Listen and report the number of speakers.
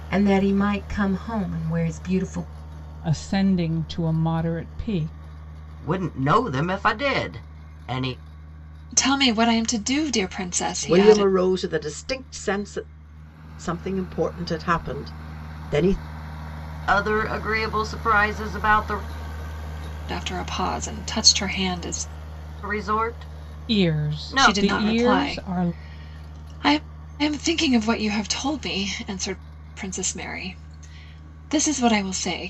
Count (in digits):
5